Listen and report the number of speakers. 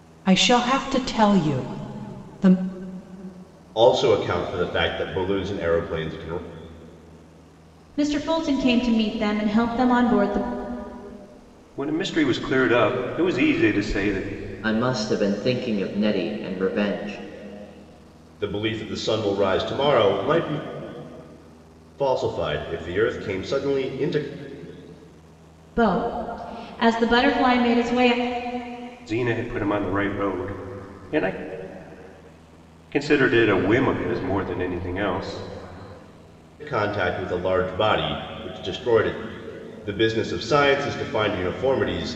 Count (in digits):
5